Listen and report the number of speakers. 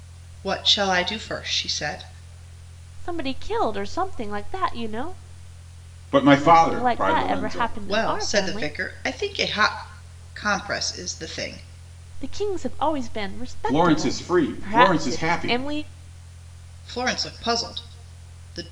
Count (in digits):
3